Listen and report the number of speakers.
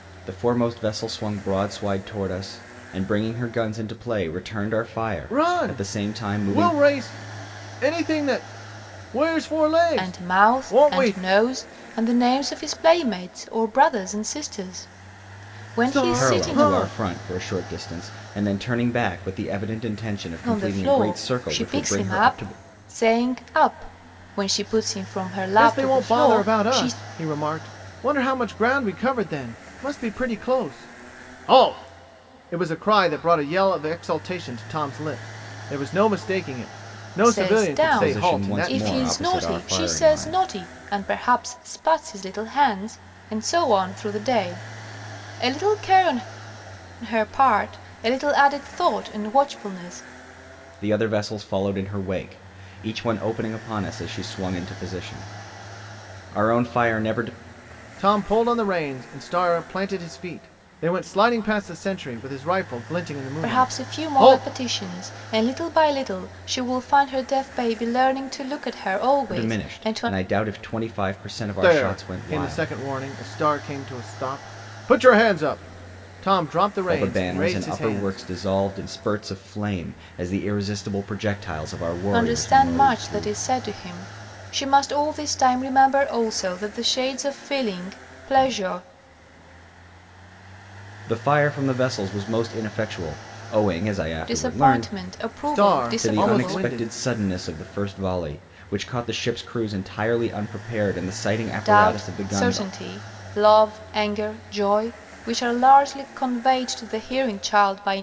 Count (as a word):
three